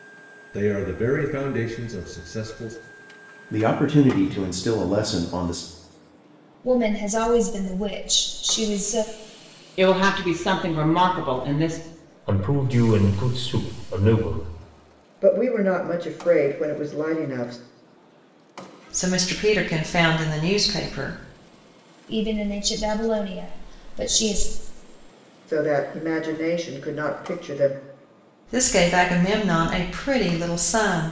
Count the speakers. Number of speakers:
seven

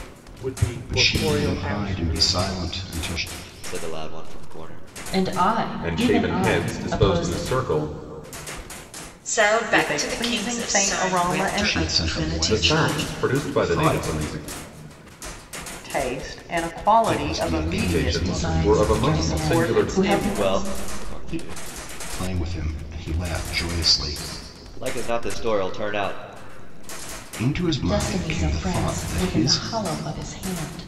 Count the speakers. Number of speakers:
eight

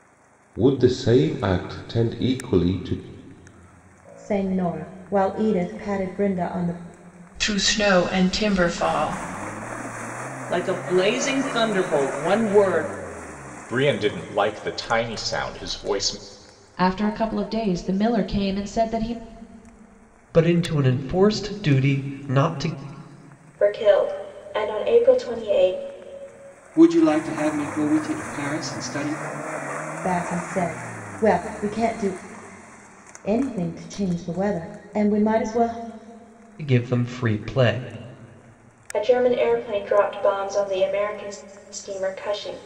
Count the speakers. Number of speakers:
nine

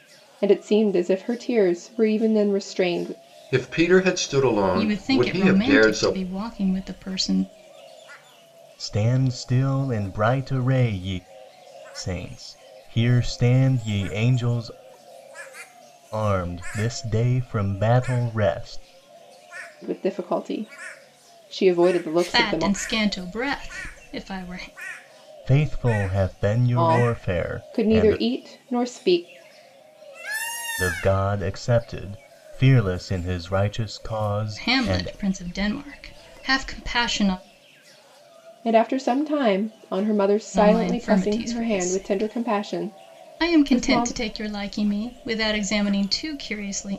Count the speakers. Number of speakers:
four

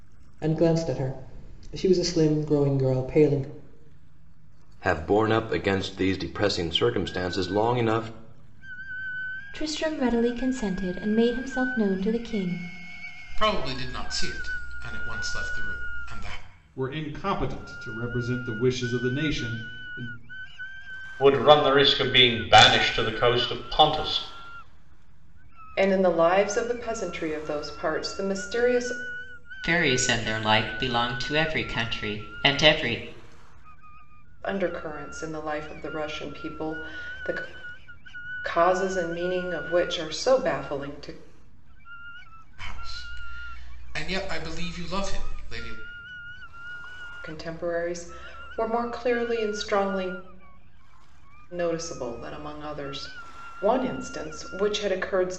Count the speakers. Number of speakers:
eight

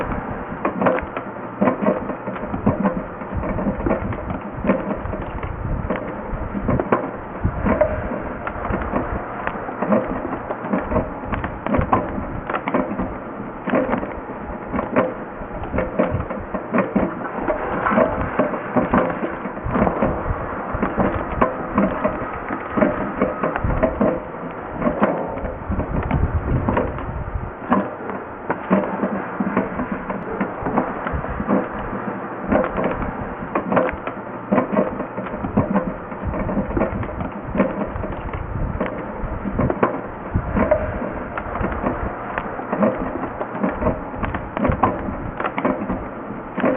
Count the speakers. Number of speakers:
zero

